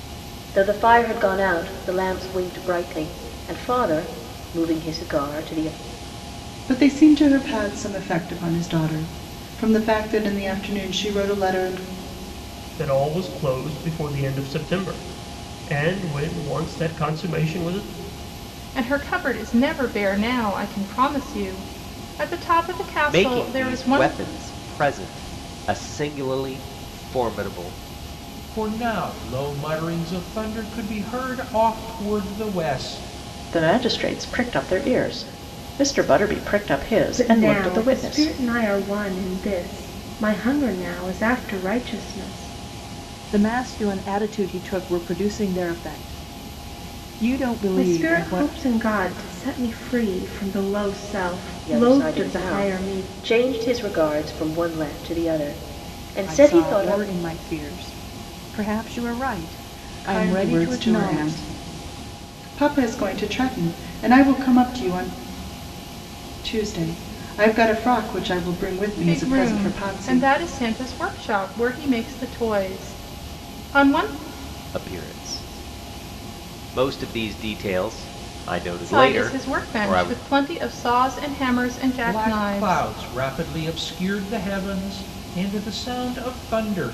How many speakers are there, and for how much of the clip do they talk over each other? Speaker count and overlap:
9, about 12%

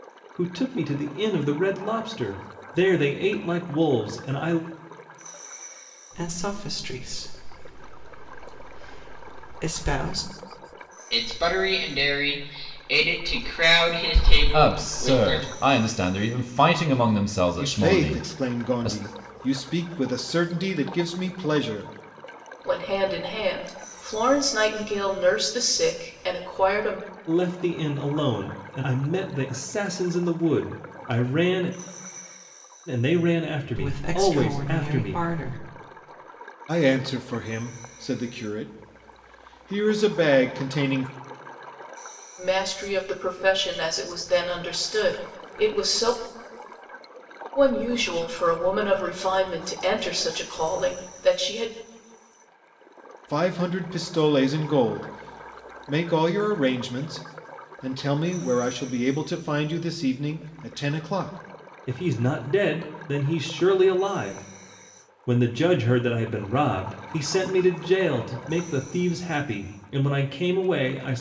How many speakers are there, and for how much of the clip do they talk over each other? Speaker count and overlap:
6, about 5%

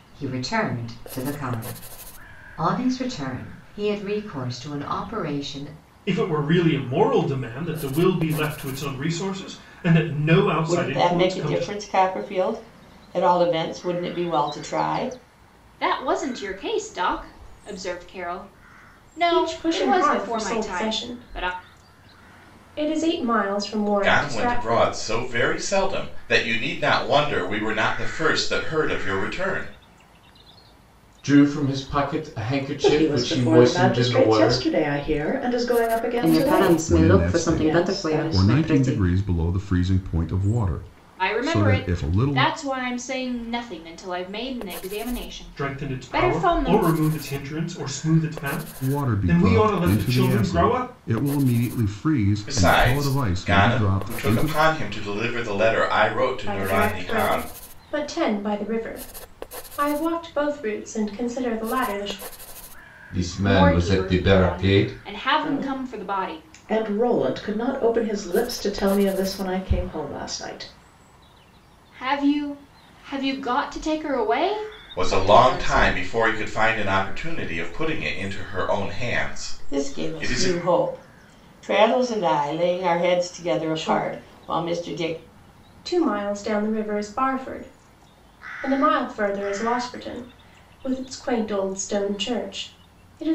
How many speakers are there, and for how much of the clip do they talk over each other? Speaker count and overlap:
10, about 25%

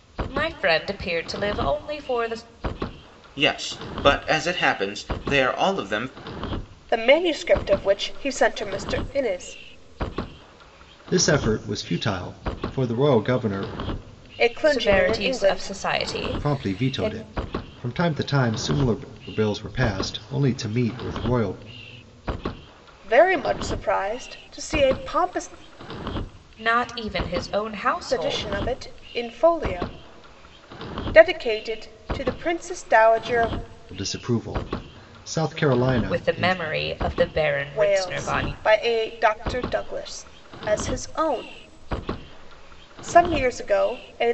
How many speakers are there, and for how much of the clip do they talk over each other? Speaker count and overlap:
4, about 9%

